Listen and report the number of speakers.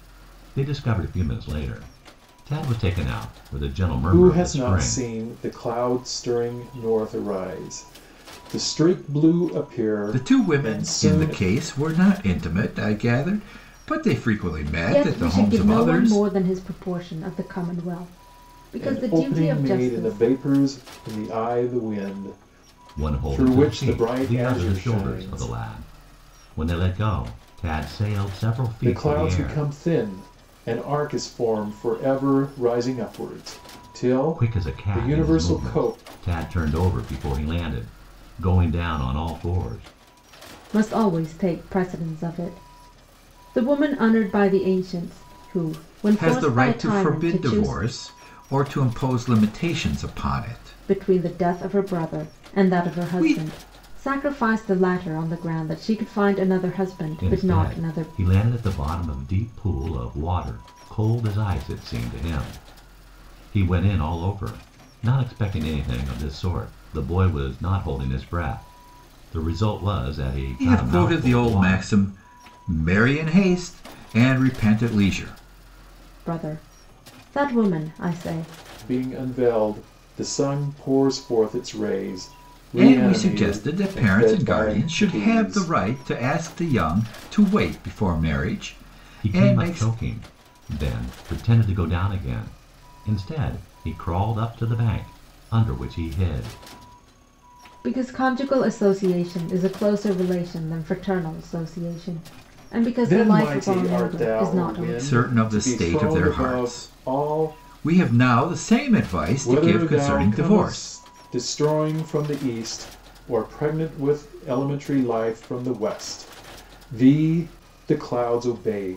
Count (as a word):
four